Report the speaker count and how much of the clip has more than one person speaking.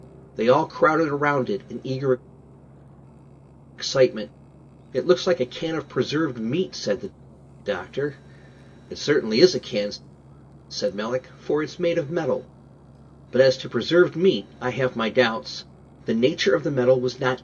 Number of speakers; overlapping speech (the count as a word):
one, no overlap